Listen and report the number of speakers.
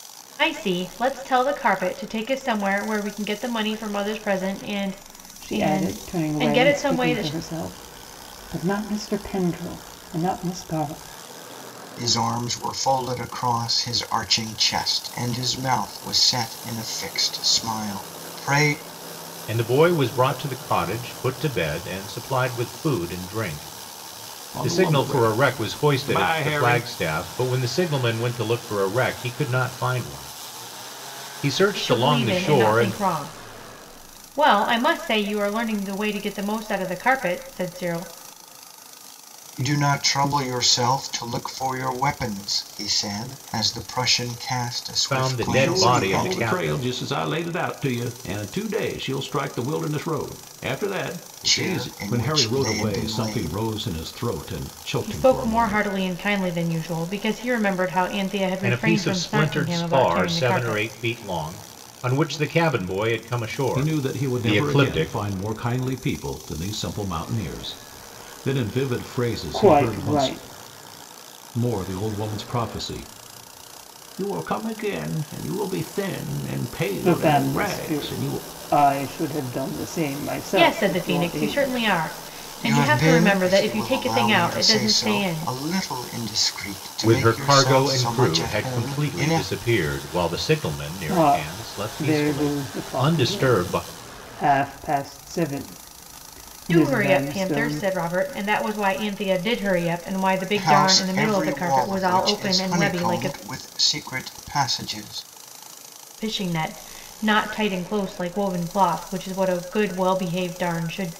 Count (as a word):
five